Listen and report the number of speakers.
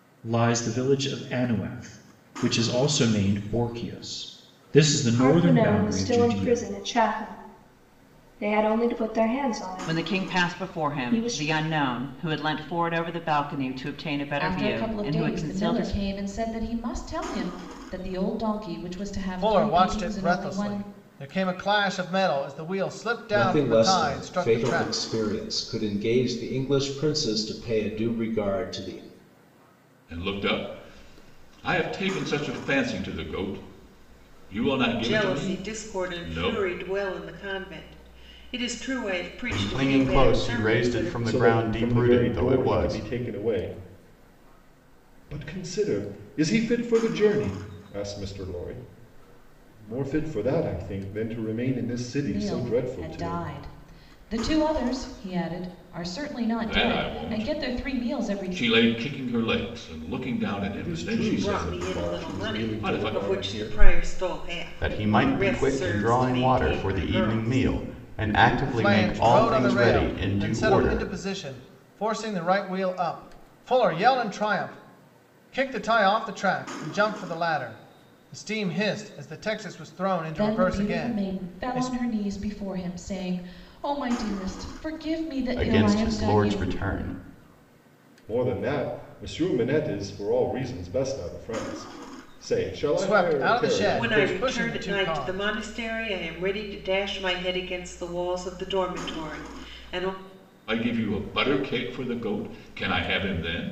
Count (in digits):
10